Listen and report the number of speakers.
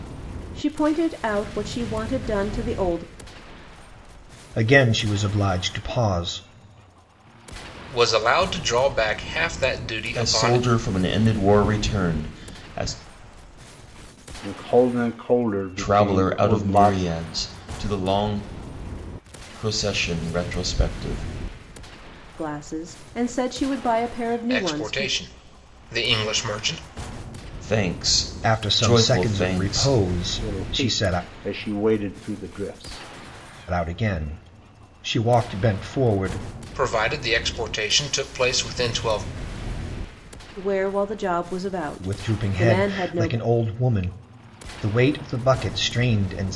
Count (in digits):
5